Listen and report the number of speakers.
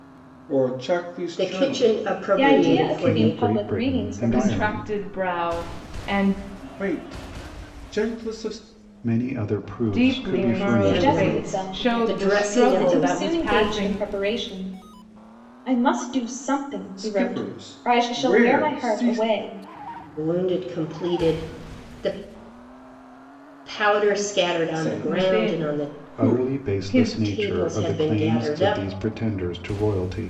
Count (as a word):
five